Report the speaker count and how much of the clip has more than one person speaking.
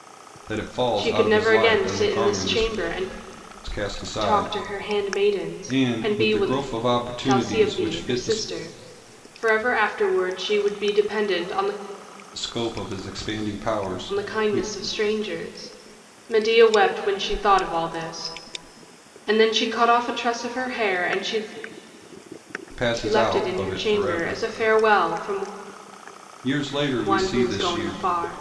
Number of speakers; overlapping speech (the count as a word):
two, about 30%